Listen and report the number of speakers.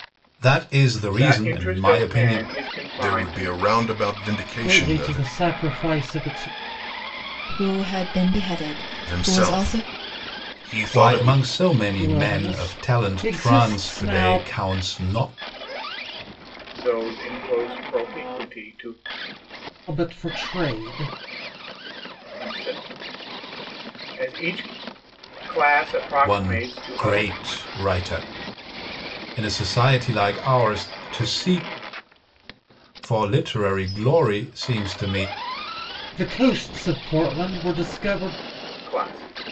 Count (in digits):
5